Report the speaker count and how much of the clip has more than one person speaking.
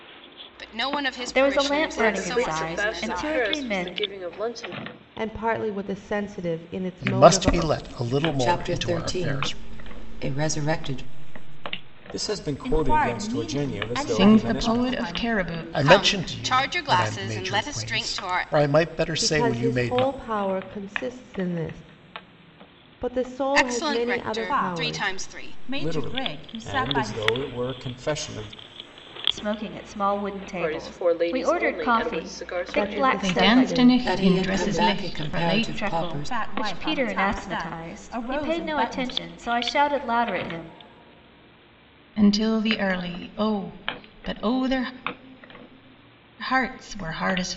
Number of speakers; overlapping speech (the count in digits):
9, about 49%